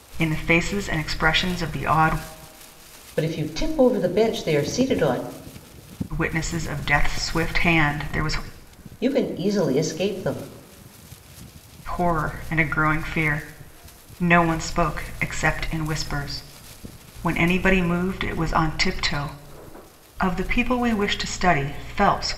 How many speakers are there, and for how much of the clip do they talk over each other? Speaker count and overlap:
2, no overlap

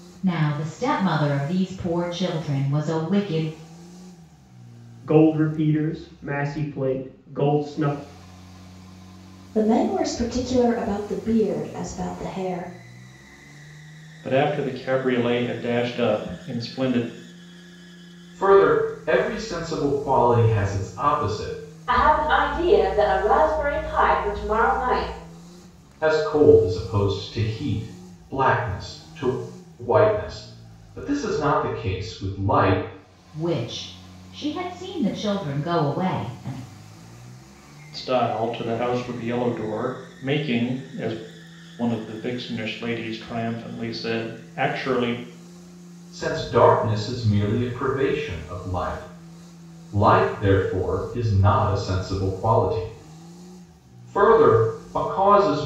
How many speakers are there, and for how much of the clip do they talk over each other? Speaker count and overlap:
6, no overlap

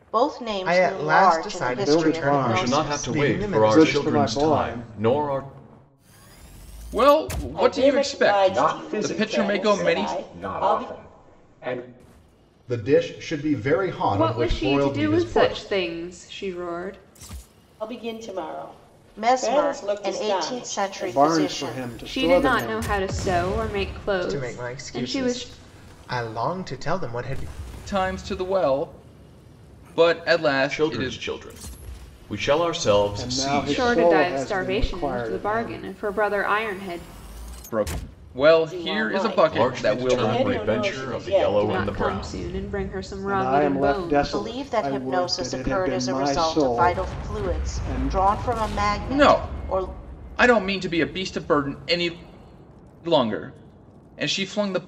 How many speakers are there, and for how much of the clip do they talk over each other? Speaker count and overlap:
9, about 48%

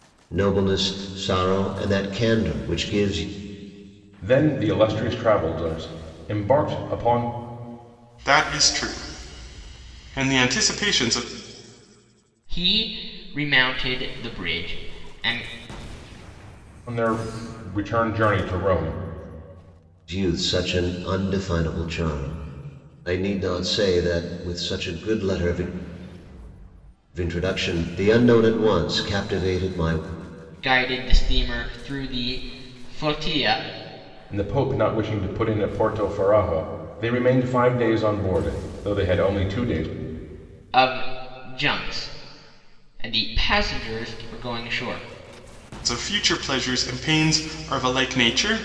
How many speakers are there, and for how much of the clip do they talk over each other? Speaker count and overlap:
4, no overlap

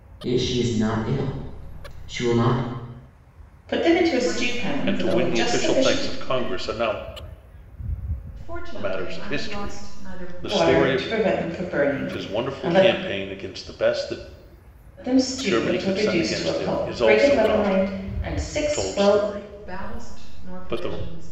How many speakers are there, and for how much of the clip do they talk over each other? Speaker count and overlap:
4, about 47%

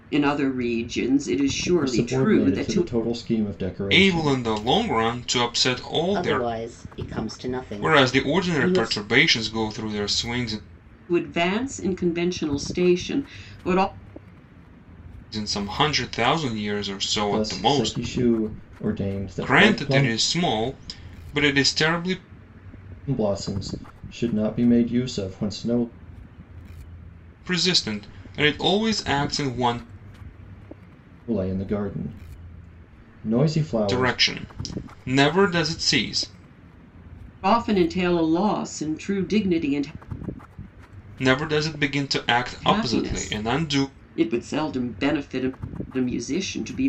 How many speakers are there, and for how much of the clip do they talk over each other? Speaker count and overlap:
4, about 14%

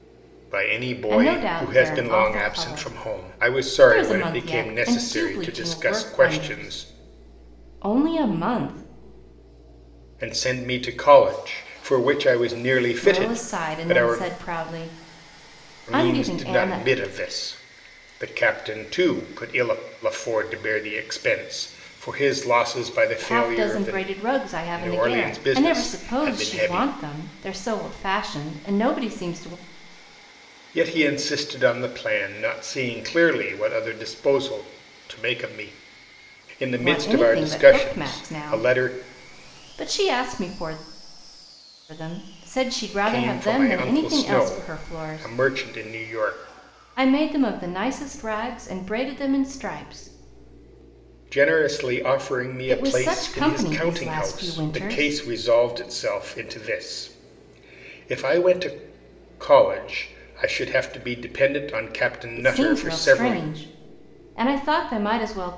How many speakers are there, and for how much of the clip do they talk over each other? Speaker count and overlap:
2, about 29%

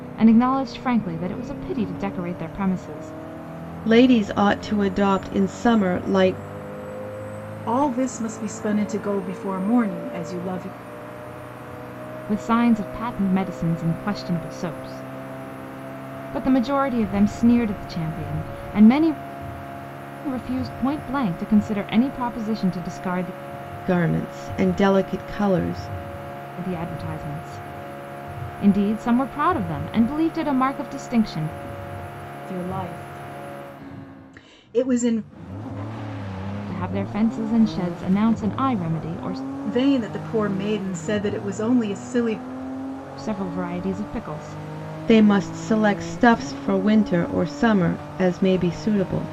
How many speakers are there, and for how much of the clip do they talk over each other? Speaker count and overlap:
3, no overlap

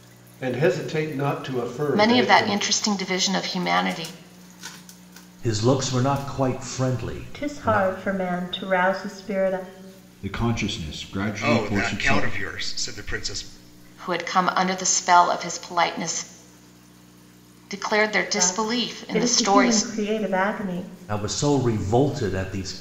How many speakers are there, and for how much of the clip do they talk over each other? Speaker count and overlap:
6, about 16%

